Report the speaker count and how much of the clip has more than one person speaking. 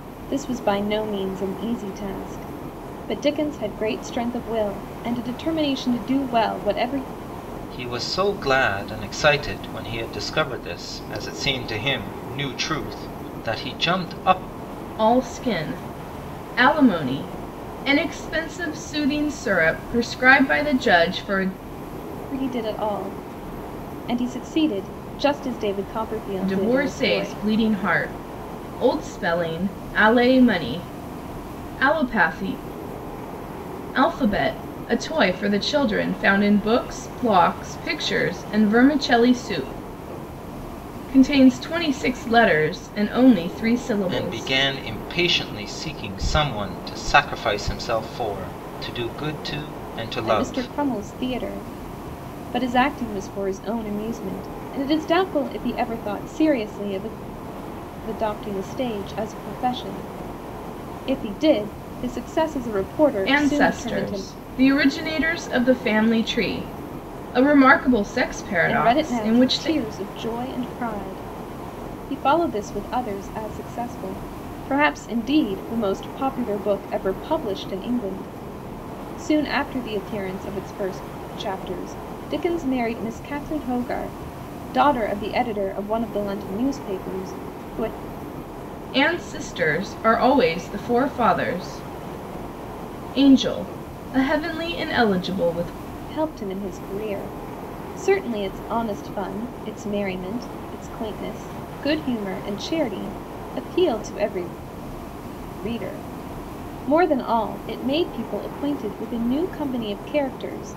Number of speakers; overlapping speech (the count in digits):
3, about 4%